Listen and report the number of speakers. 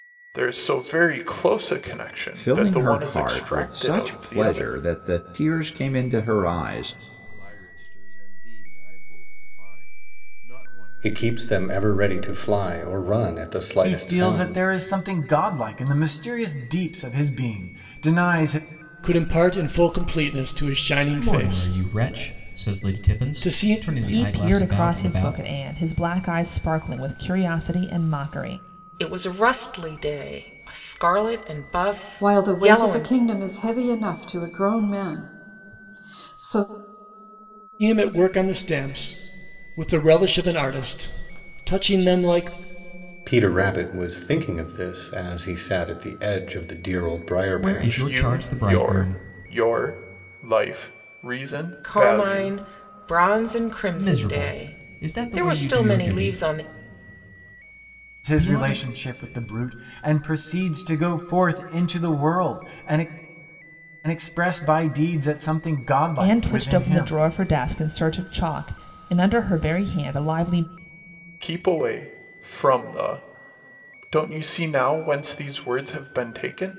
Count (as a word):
ten